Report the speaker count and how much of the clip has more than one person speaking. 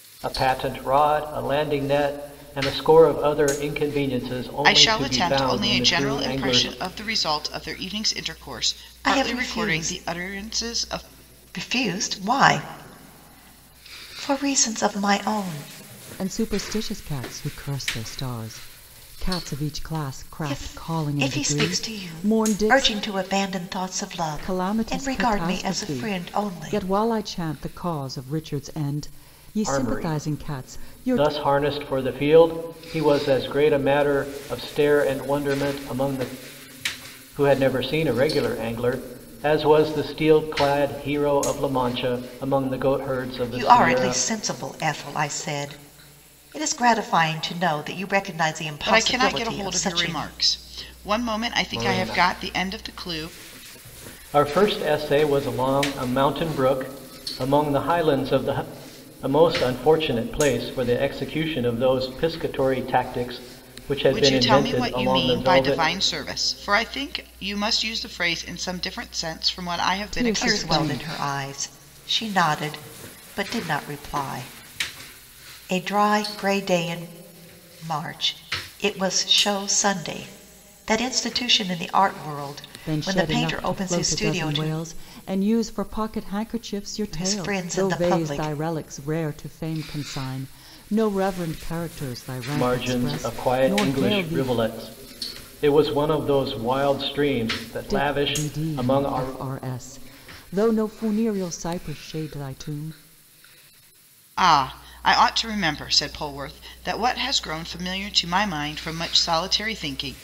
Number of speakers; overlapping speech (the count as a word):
four, about 22%